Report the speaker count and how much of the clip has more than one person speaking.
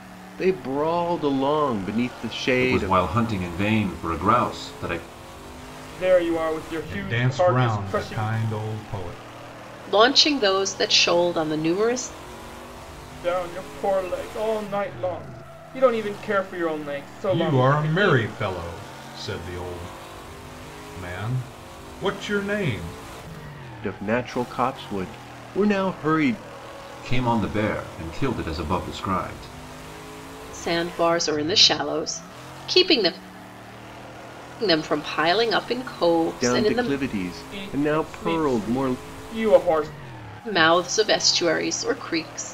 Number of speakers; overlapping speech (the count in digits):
5, about 12%